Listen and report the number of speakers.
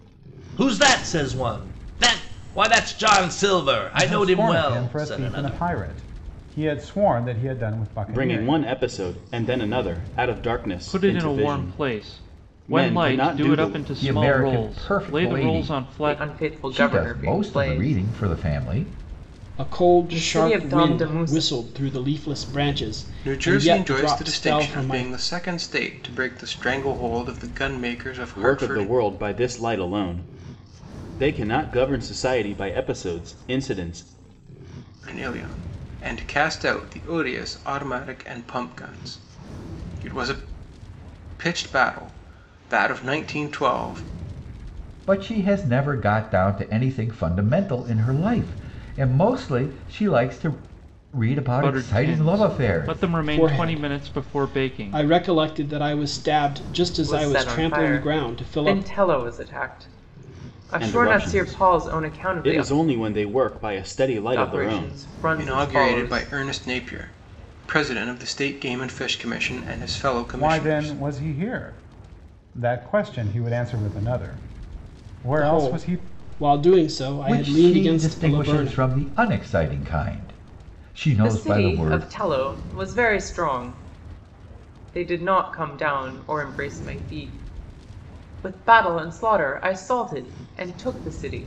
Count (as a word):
eight